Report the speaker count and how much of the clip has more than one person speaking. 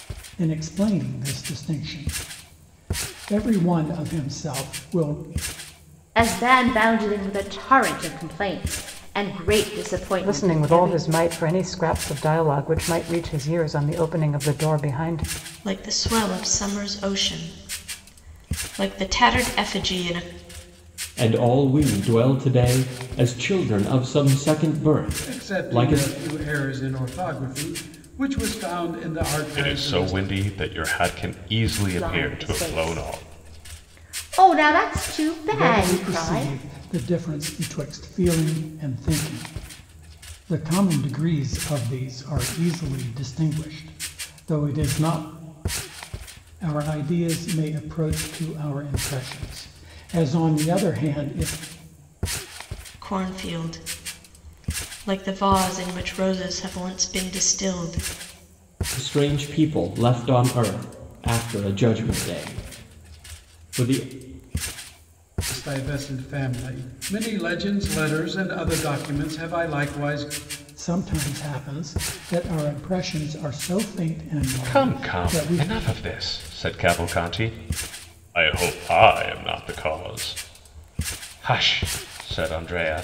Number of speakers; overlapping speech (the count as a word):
seven, about 7%